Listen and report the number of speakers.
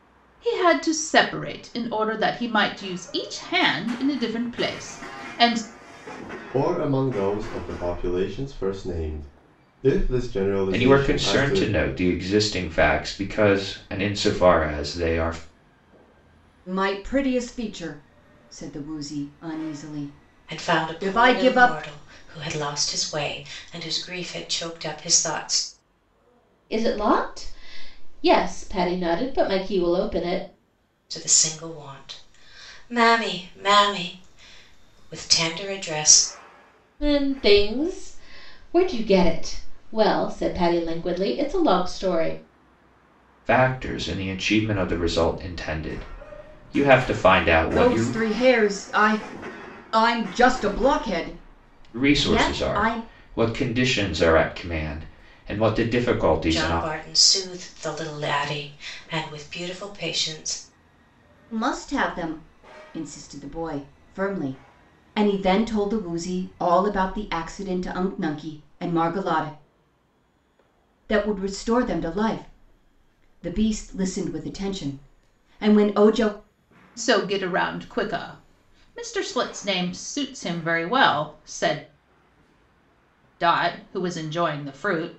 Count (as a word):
six